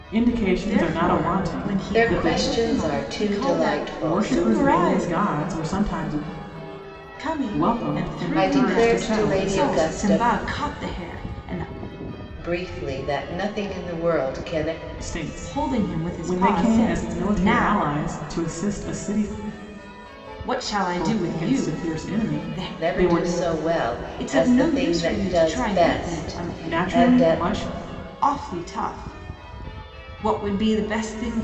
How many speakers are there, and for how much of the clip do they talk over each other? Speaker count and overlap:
three, about 49%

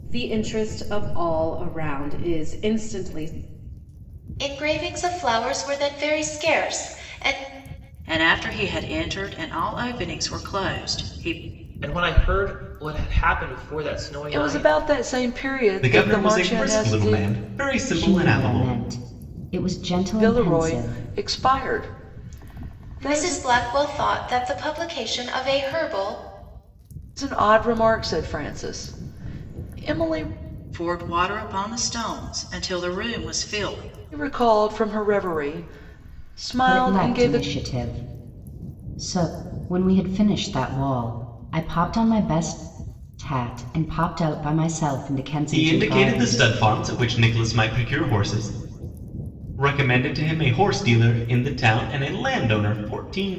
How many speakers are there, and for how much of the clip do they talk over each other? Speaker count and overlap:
seven, about 11%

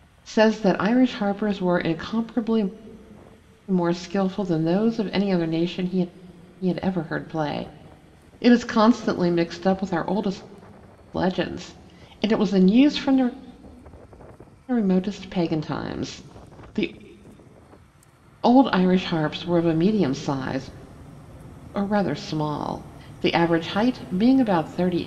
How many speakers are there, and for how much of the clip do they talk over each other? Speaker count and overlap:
one, no overlap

